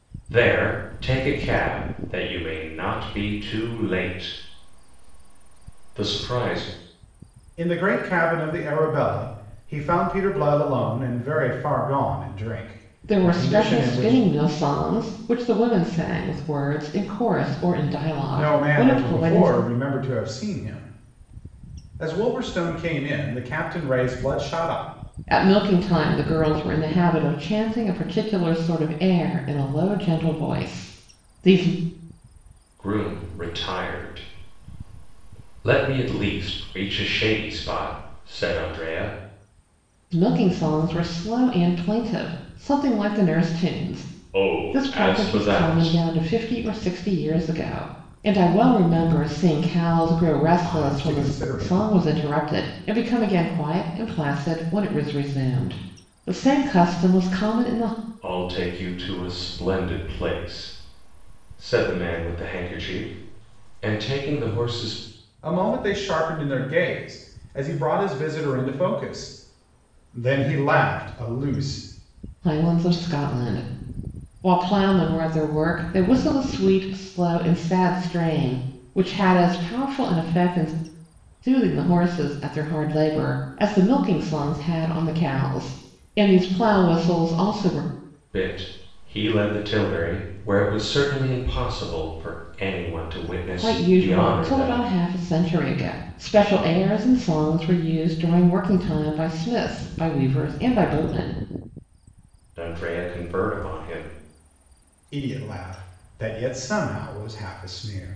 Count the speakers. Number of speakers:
three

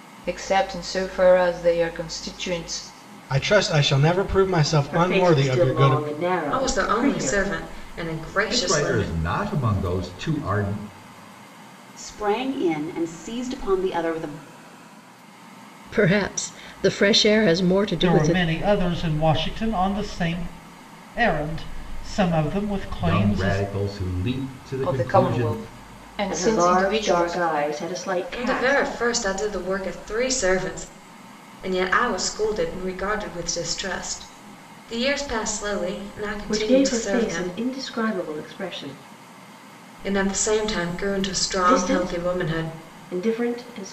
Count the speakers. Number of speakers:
eight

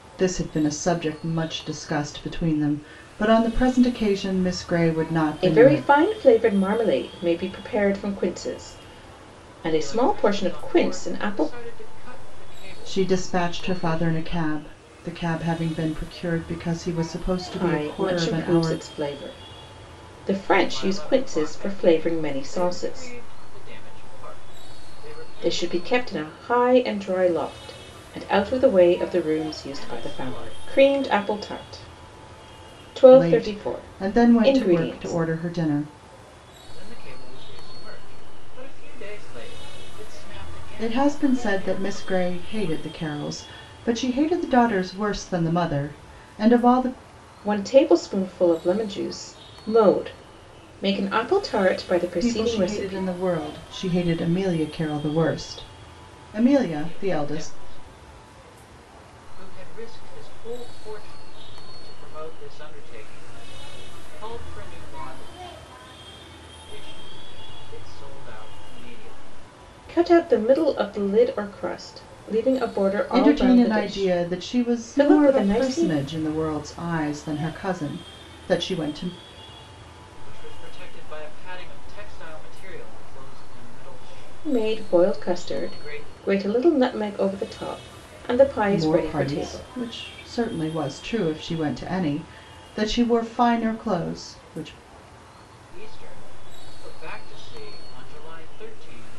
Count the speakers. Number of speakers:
three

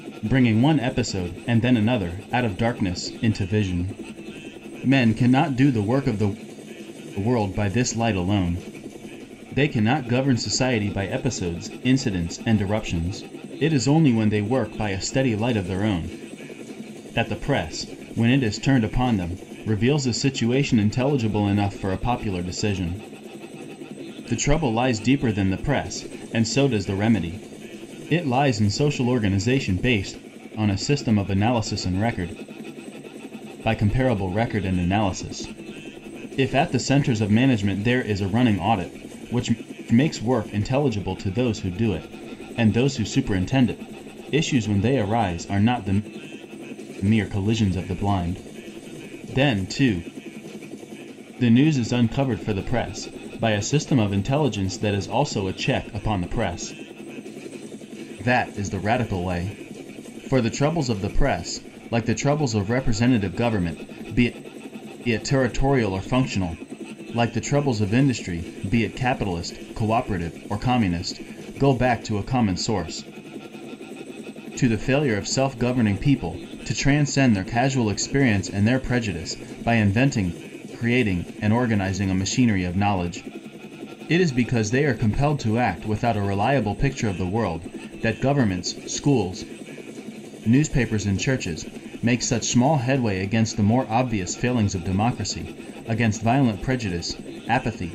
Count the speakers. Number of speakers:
one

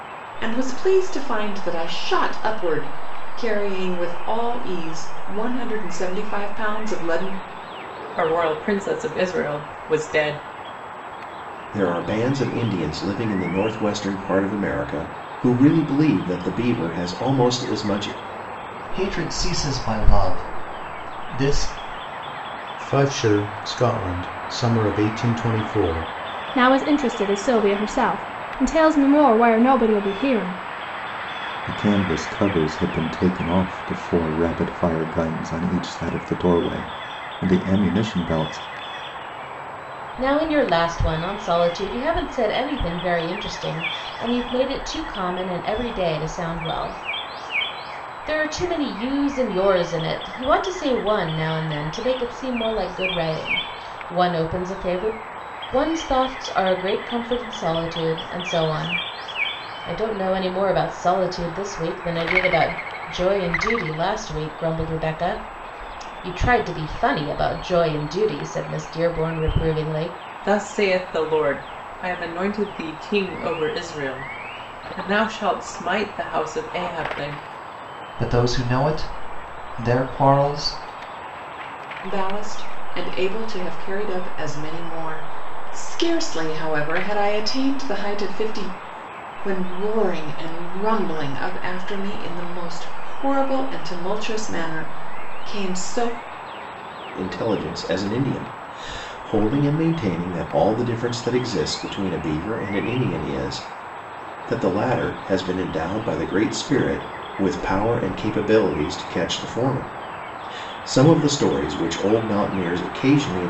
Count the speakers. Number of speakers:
eight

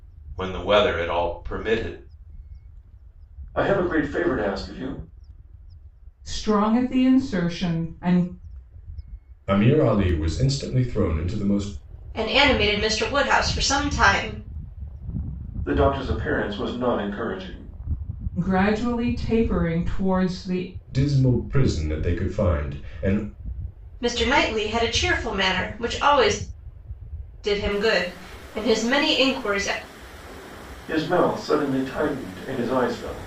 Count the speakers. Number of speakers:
five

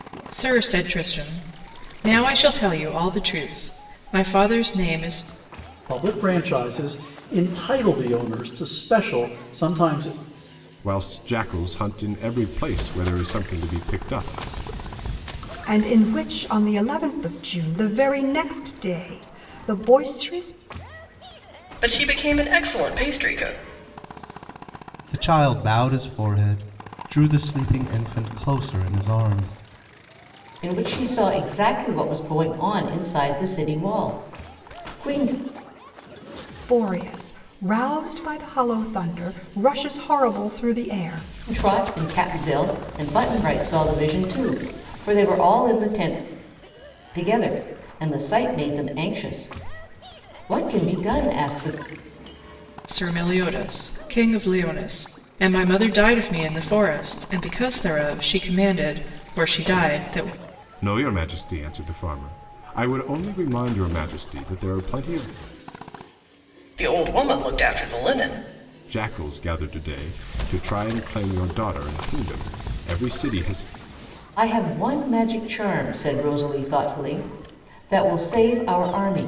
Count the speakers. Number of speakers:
seven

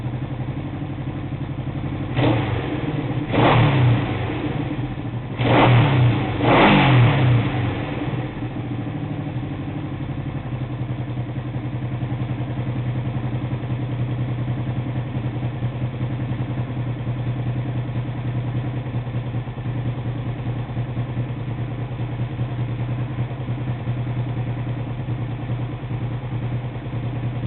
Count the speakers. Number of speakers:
zero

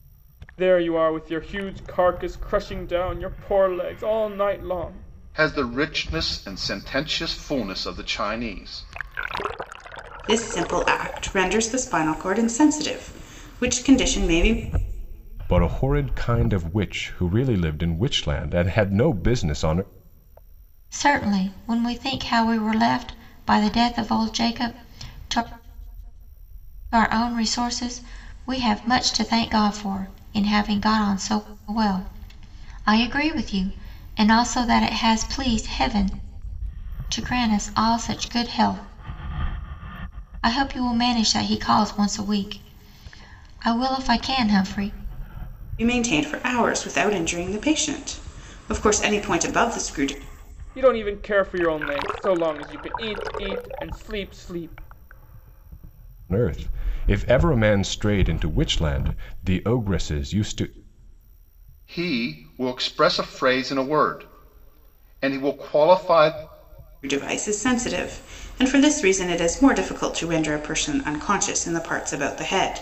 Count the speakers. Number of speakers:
five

